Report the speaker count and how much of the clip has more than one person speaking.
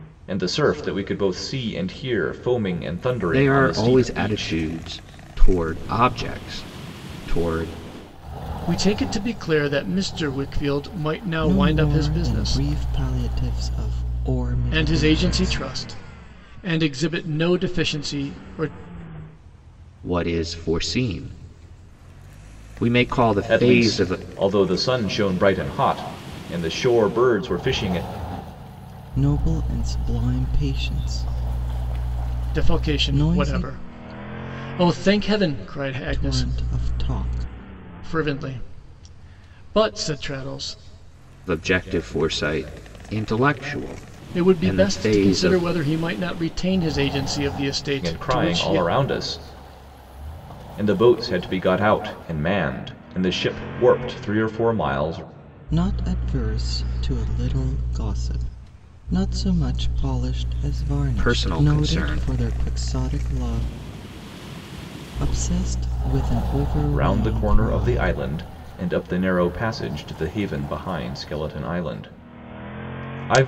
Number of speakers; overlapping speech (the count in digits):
4, about 14%